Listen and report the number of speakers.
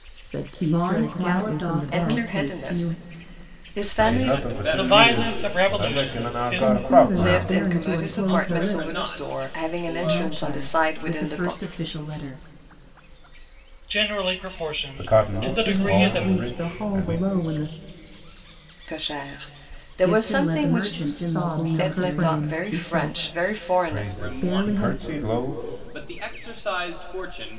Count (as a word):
six